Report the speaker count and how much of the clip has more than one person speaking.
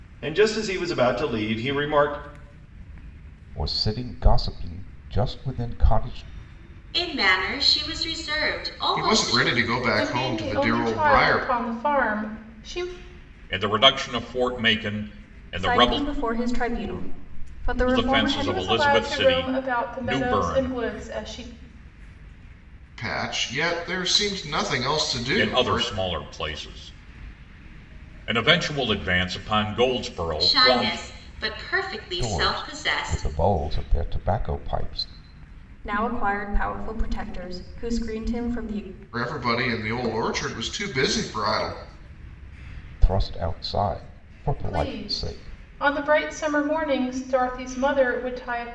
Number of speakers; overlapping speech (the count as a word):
seven, about 18%